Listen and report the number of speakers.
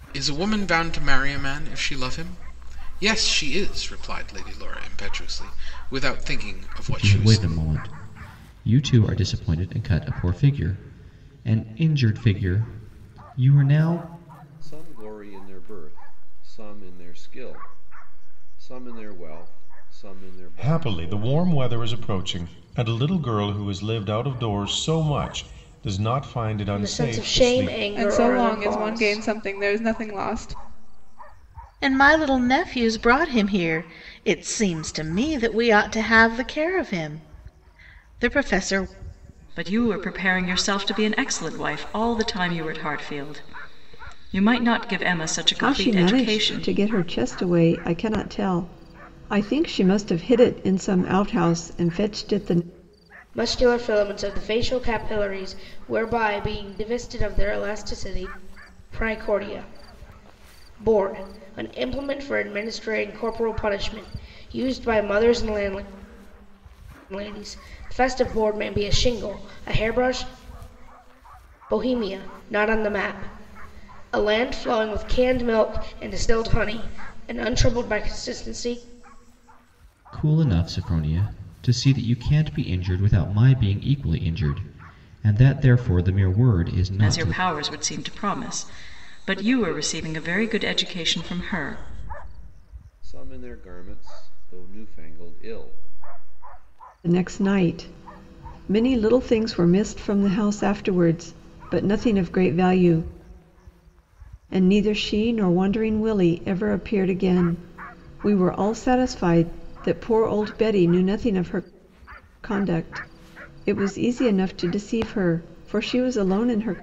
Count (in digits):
9